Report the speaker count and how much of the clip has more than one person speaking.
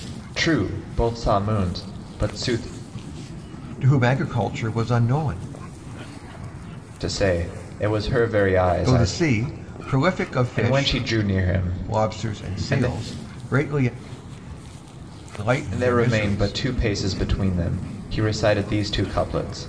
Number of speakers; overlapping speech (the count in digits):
2, about 14%